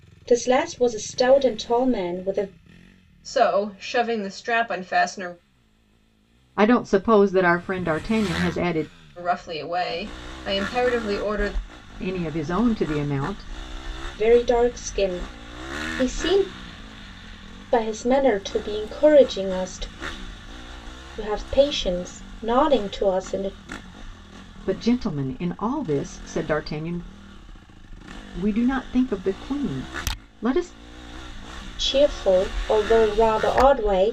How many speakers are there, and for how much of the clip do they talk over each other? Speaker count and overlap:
three, no overlap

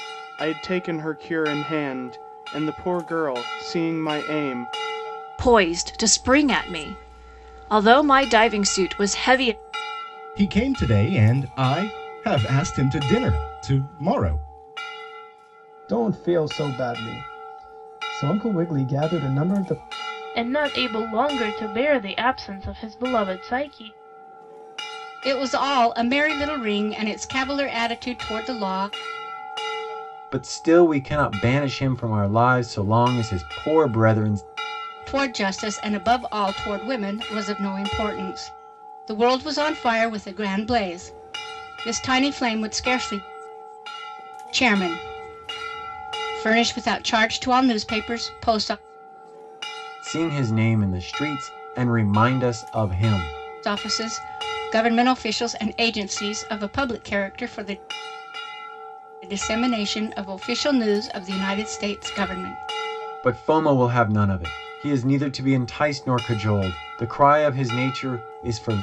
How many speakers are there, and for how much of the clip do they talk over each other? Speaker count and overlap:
seven, no overlap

